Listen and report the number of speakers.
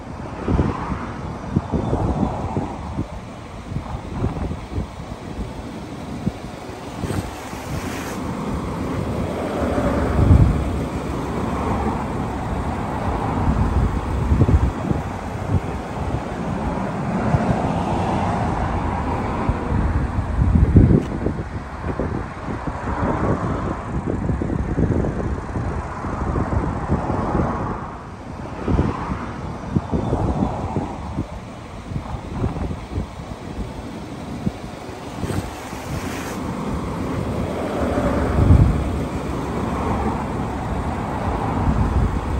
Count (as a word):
zero